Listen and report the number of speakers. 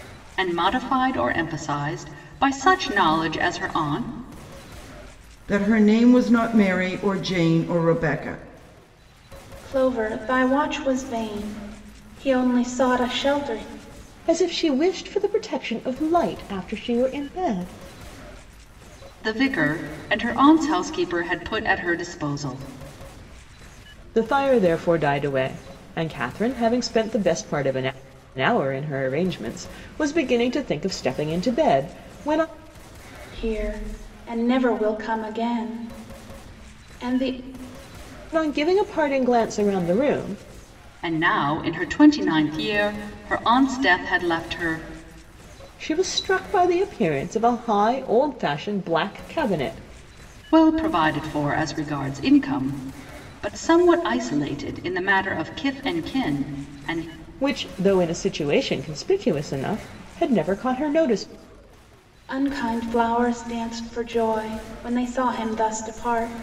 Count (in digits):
4